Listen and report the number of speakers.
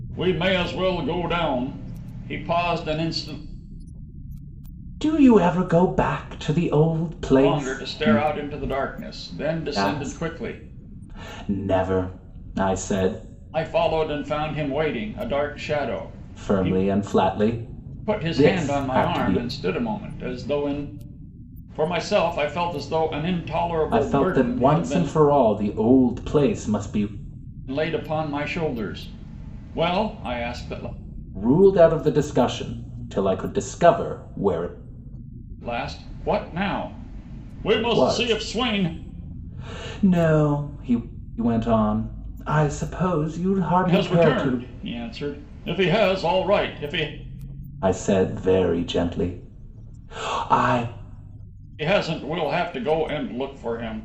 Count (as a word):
two